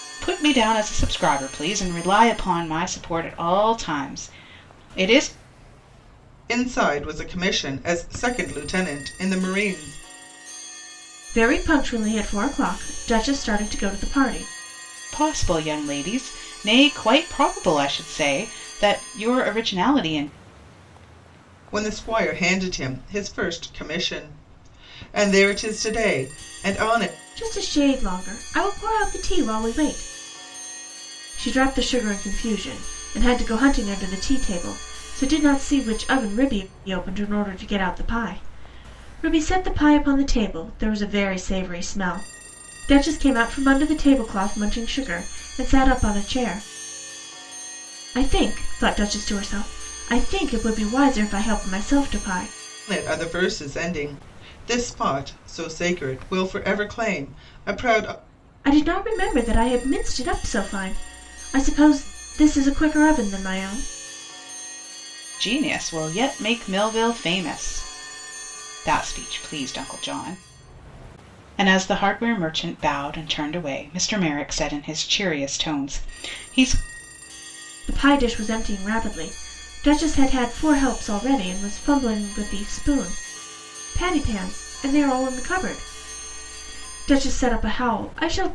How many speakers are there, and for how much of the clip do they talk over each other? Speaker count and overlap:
three, no overlap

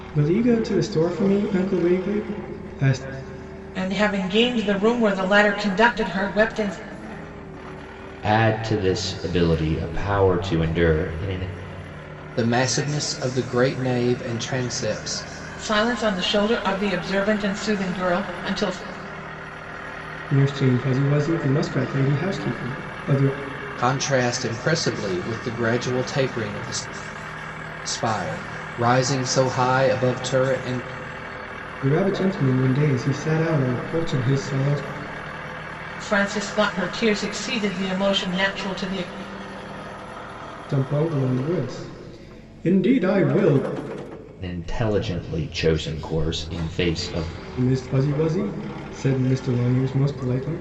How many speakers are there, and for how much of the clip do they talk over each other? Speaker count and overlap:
four, no overlap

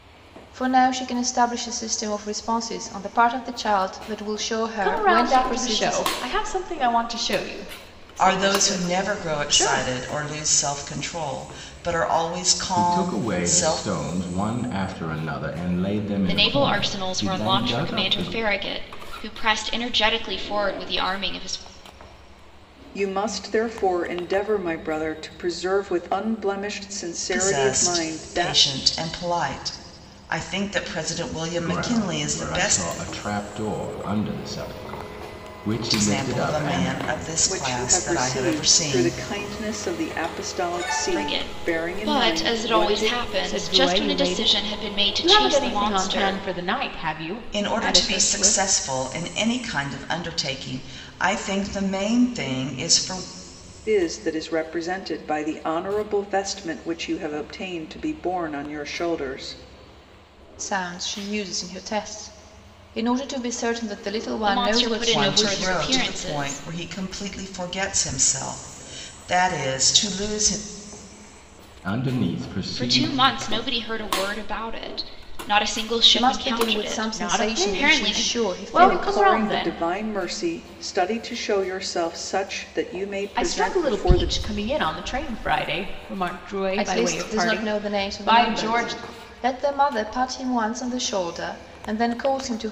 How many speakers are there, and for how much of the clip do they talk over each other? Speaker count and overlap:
six, about 30%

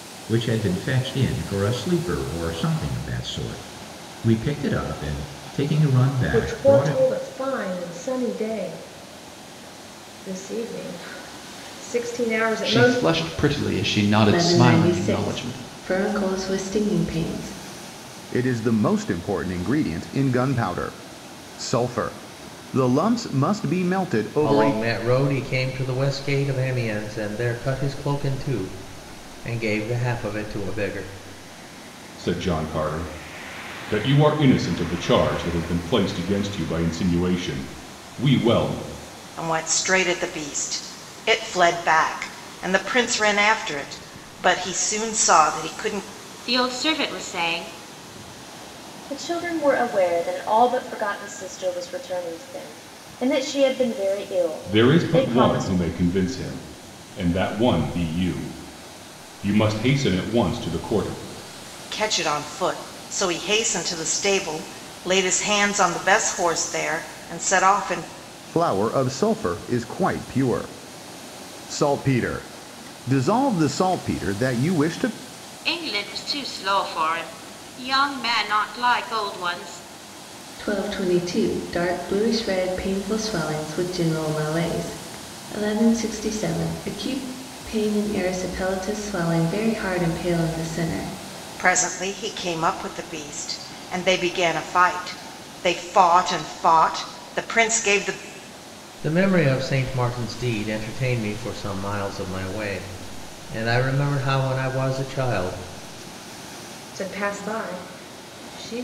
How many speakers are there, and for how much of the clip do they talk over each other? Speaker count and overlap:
ten, about 4%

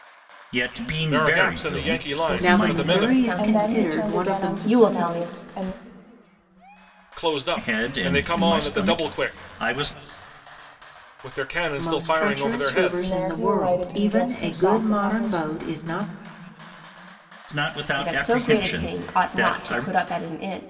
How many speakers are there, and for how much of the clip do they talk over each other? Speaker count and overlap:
five, about 56%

